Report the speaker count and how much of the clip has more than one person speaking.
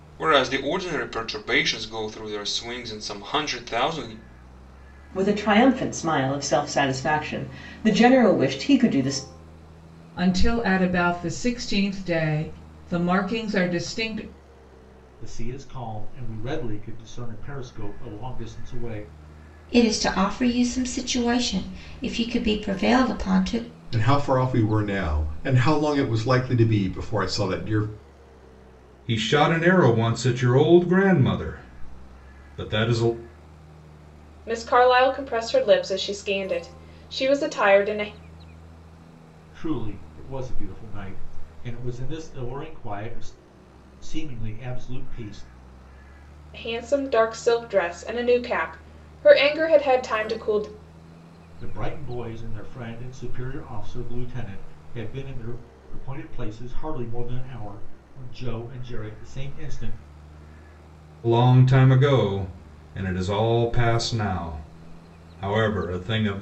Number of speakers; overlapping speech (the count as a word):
eight, no overlap